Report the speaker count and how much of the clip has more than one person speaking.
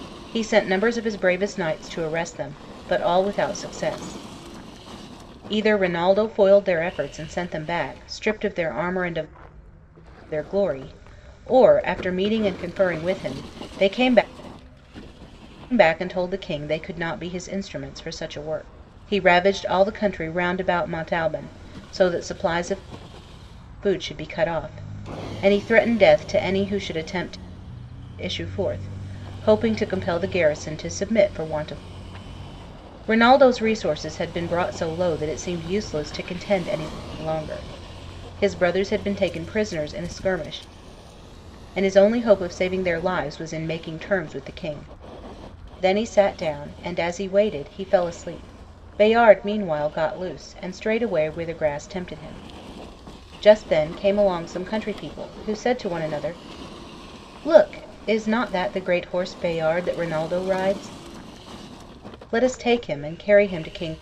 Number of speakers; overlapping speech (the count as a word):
one, no overlap